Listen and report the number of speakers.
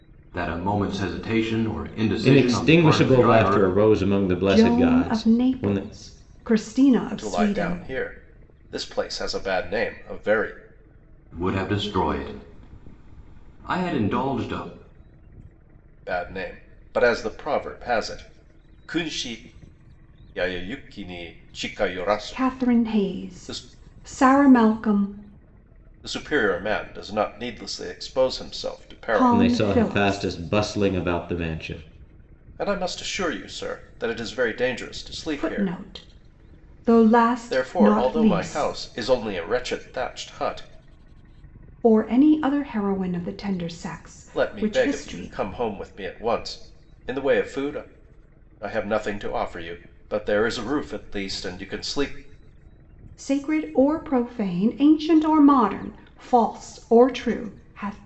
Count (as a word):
four